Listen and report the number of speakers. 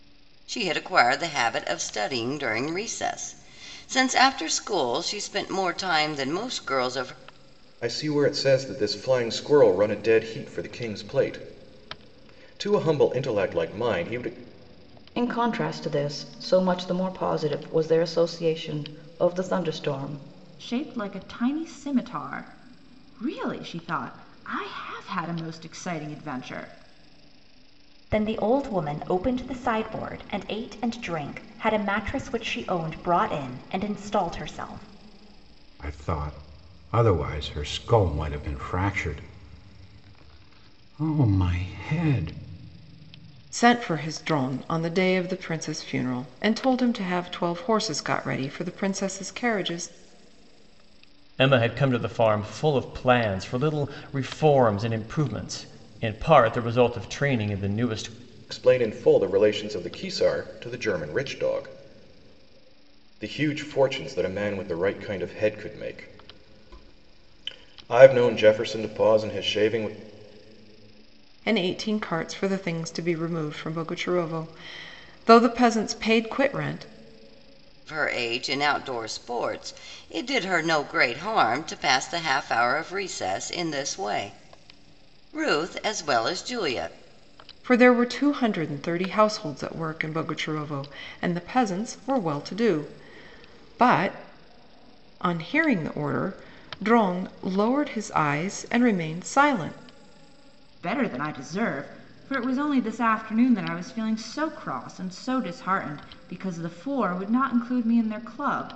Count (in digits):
8